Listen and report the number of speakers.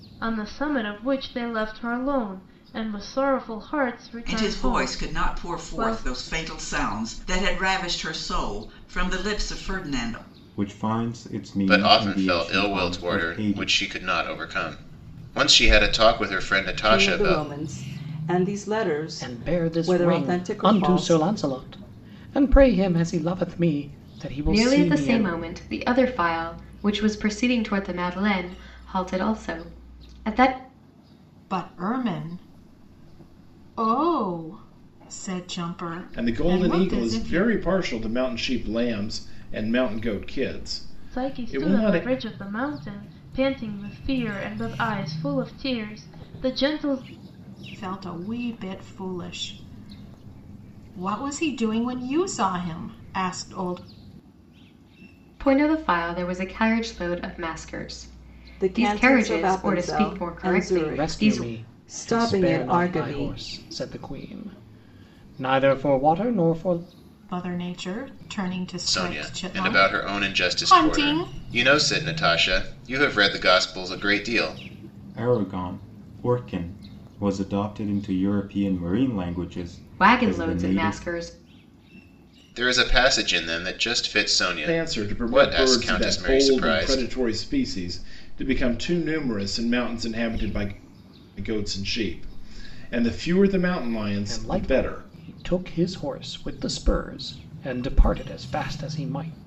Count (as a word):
nine